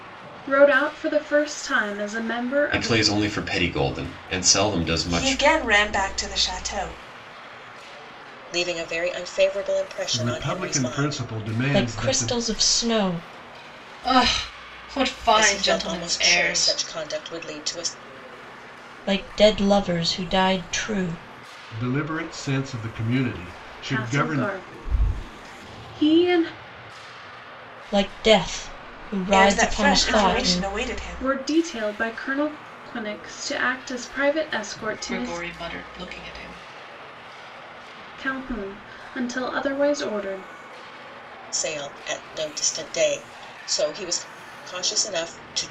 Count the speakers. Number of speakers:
7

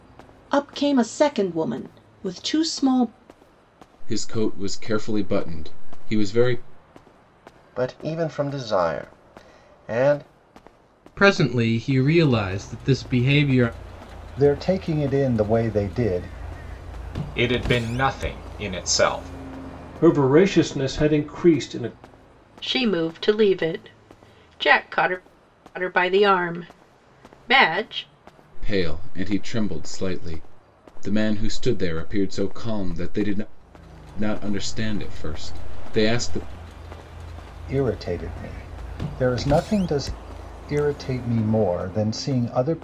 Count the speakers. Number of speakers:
8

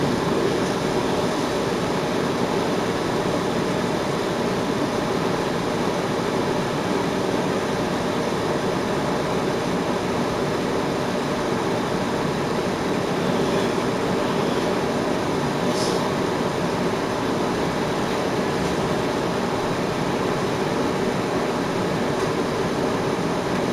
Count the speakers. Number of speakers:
0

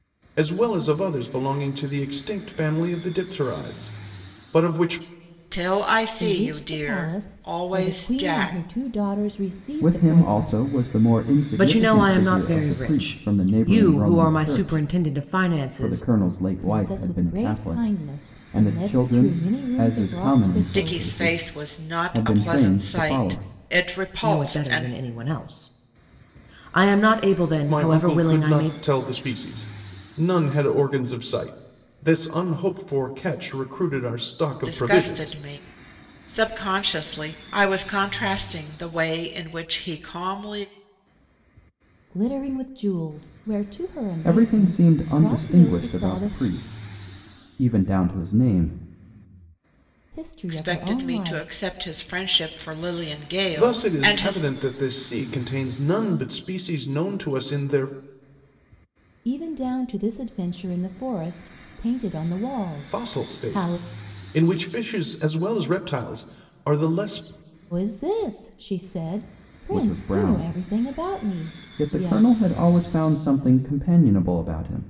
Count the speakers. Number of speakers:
5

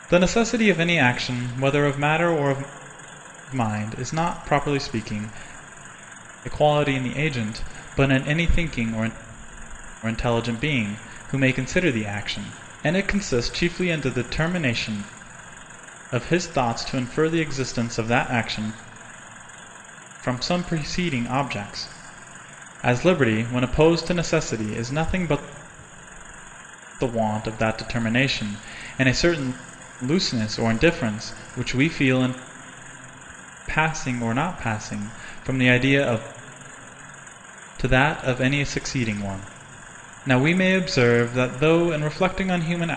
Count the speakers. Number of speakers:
1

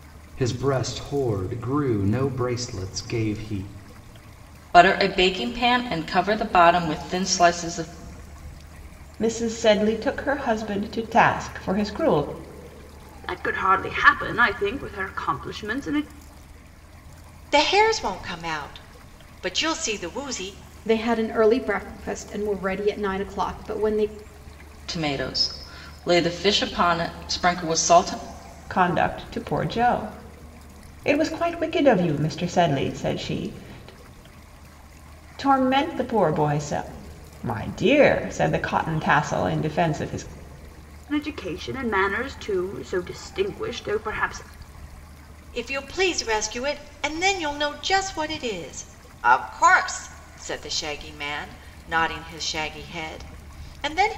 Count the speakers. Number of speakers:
6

